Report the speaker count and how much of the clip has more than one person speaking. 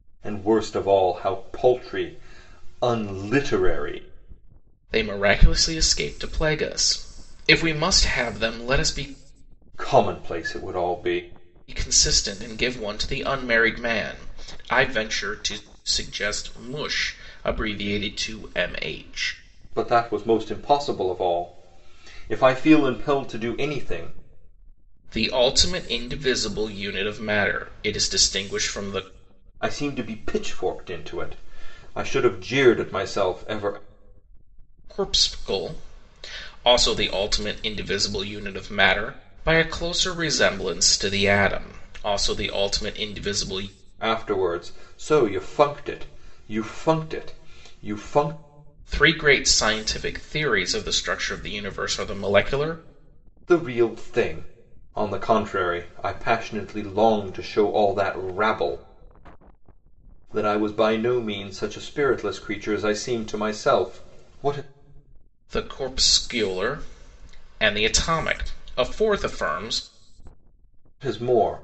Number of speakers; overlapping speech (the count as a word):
two, no overlap